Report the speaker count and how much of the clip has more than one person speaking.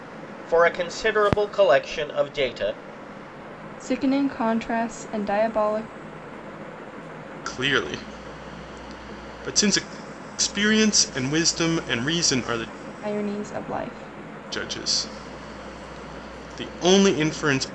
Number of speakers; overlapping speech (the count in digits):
3, no overlap